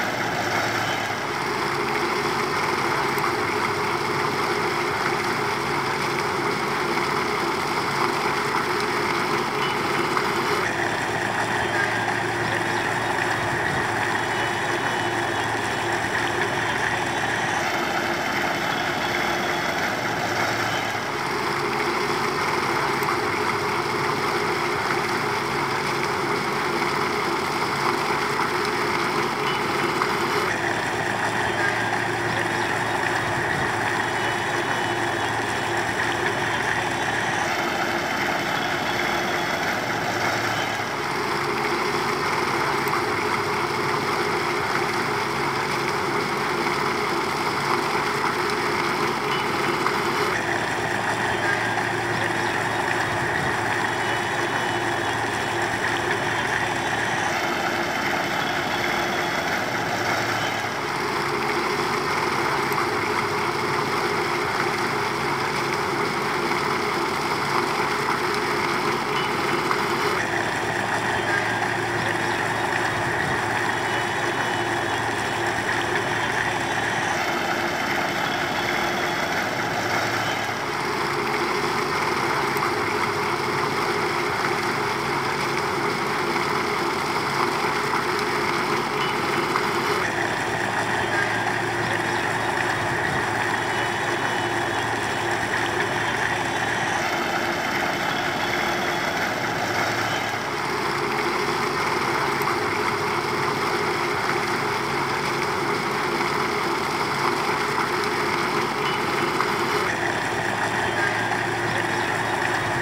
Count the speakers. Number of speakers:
zero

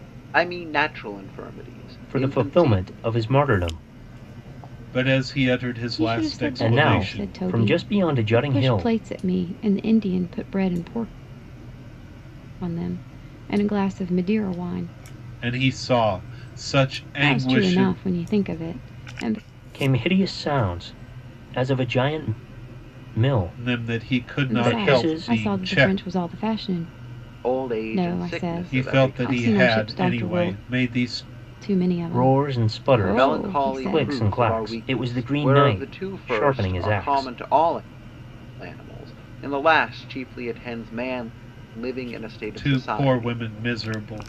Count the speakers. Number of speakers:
four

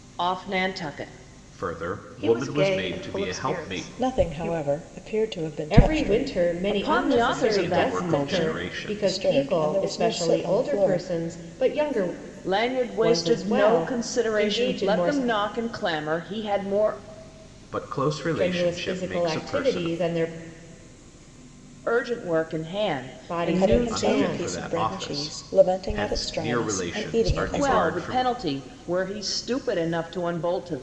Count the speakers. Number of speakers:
five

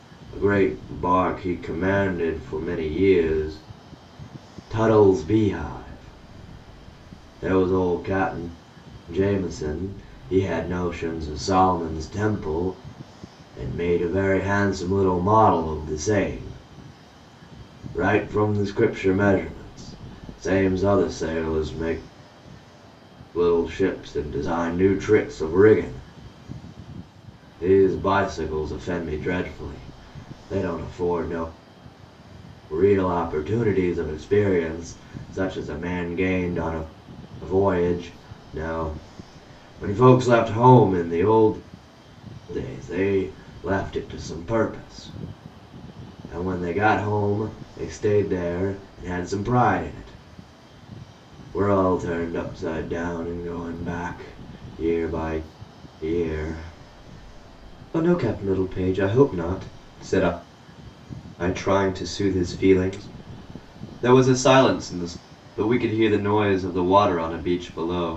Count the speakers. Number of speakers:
one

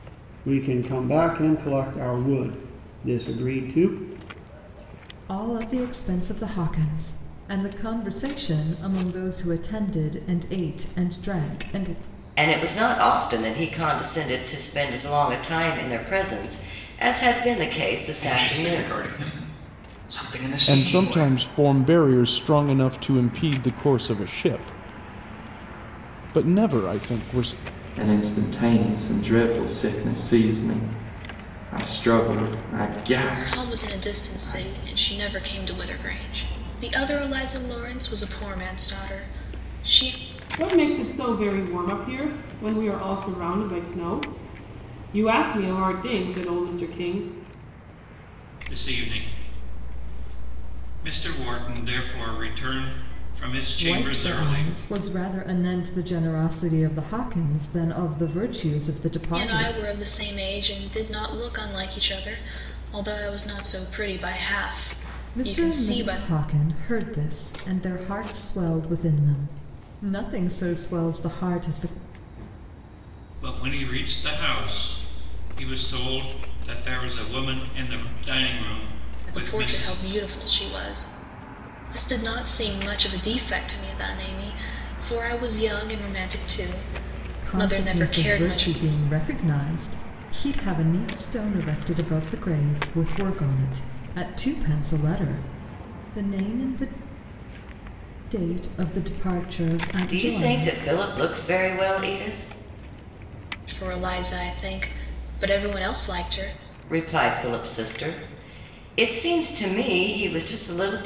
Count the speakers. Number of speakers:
nine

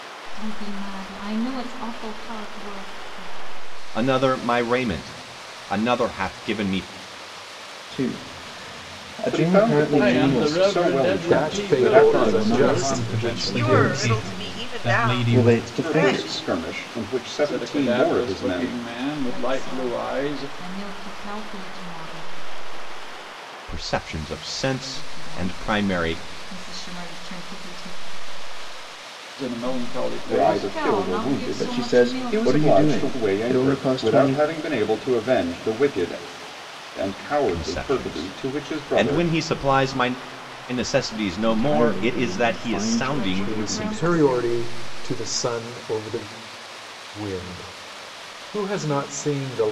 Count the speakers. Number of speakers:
nine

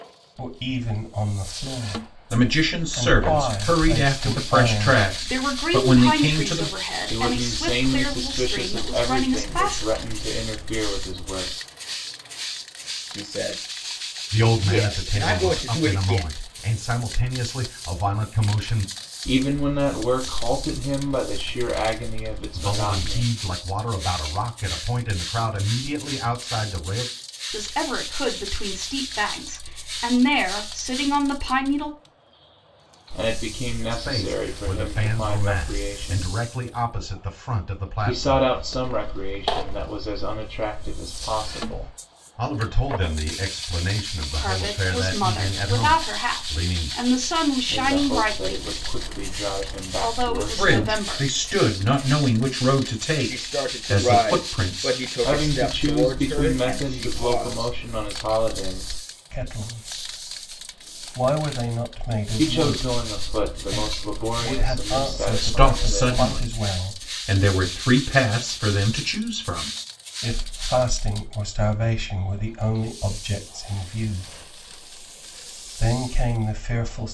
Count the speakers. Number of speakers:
six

